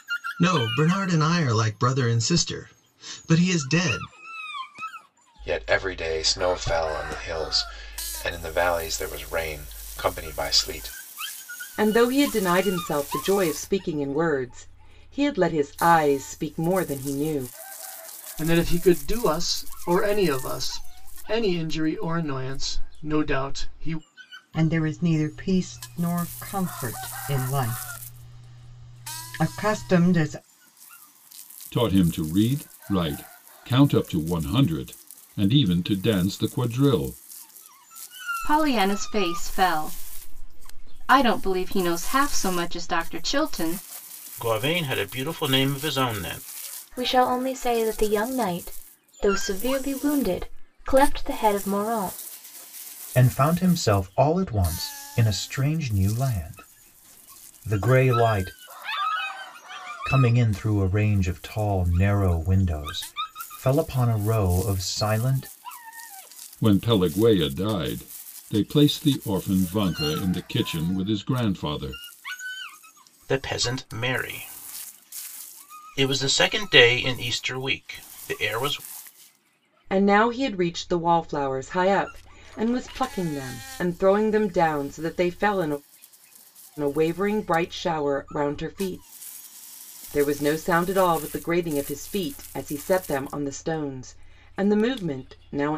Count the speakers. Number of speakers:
ten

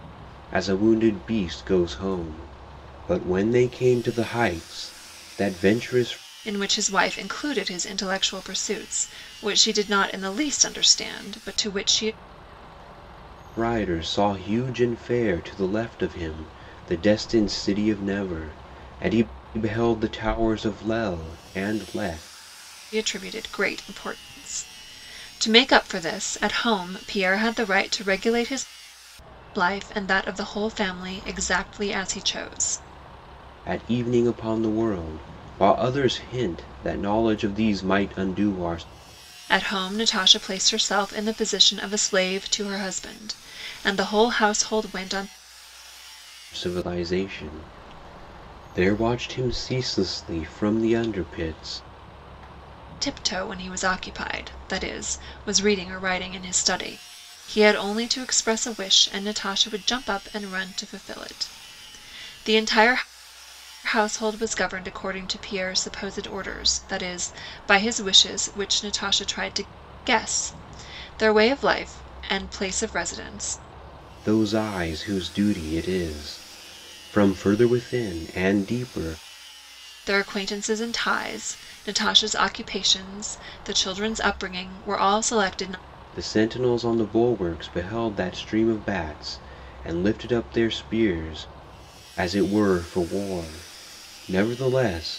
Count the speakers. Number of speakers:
two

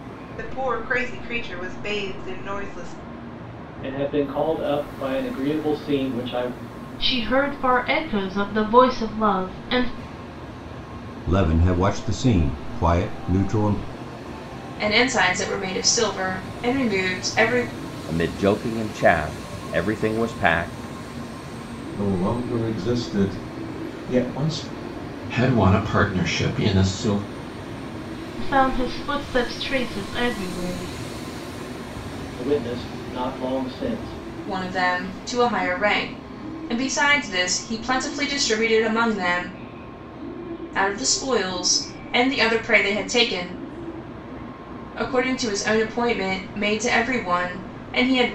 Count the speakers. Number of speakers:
eight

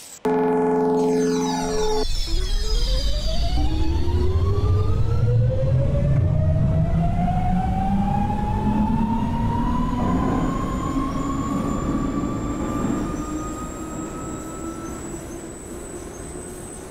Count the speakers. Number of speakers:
zero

